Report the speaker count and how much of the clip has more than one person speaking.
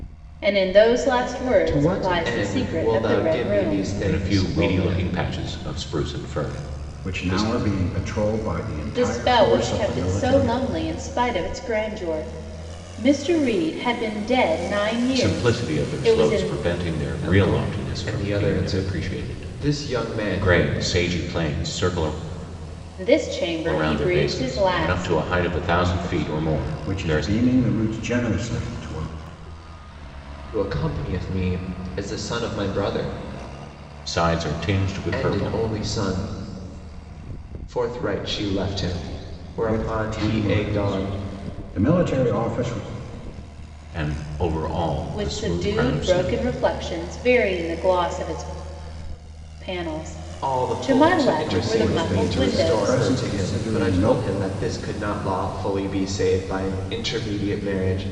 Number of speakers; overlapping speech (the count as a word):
four, about 35%